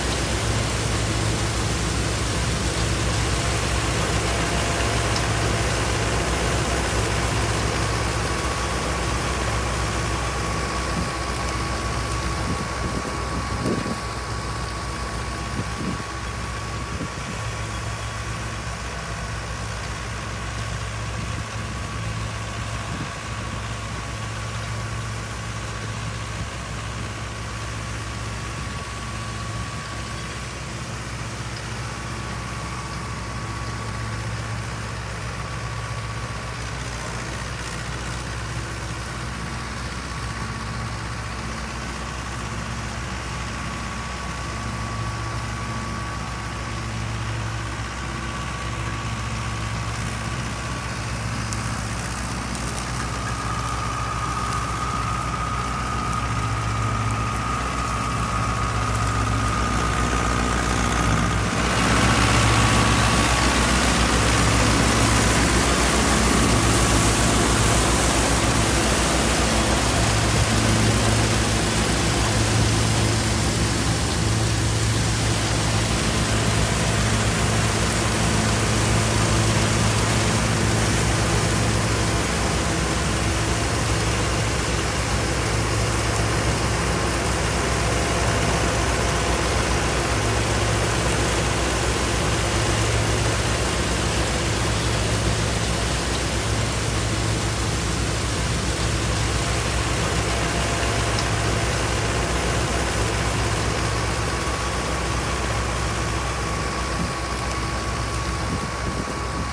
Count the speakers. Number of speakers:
0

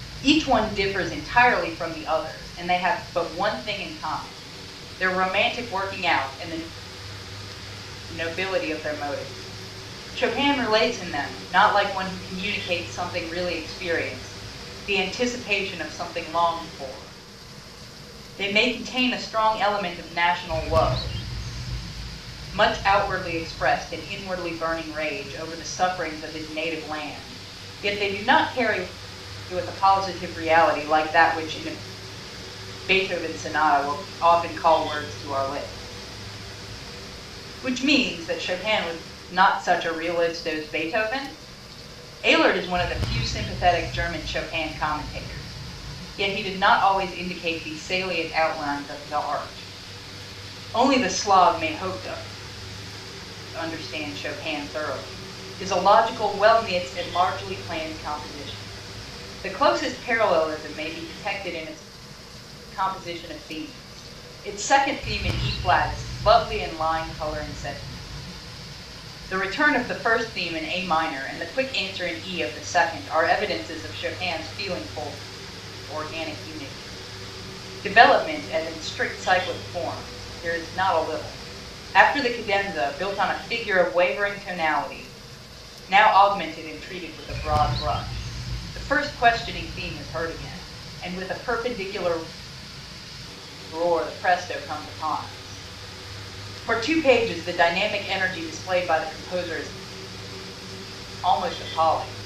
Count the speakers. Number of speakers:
1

